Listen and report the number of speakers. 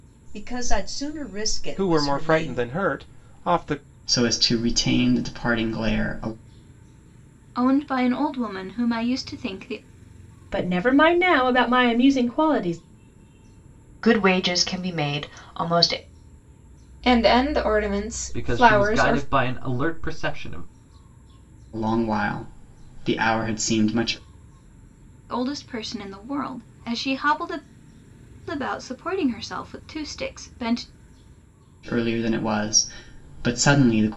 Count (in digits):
8